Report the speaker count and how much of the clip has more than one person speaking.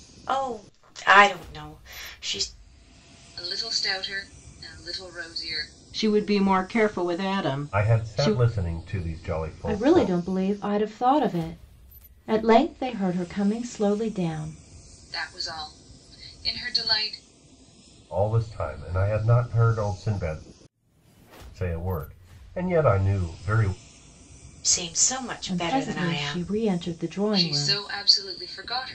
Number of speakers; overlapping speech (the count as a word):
five, about 9%